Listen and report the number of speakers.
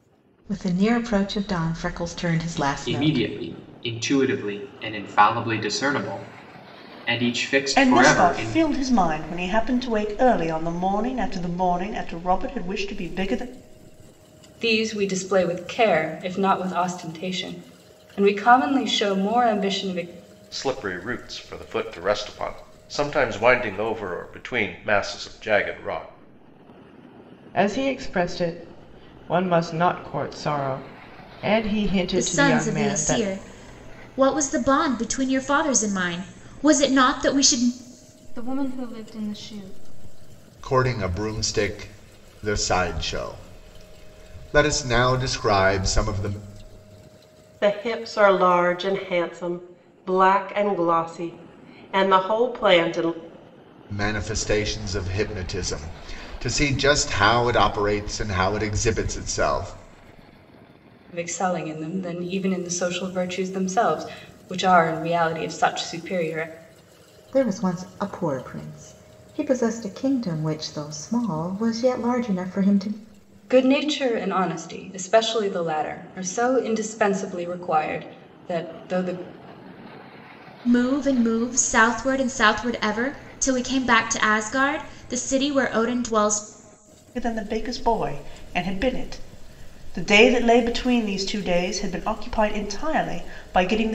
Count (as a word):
ten